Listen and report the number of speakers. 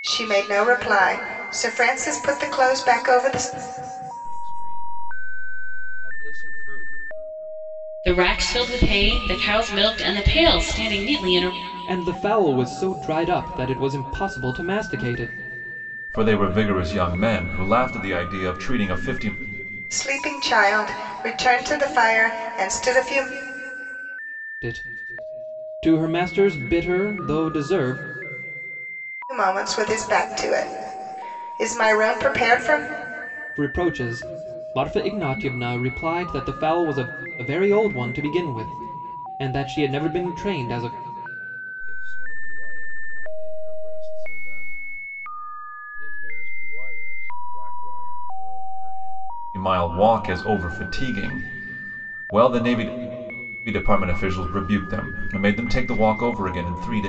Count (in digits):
5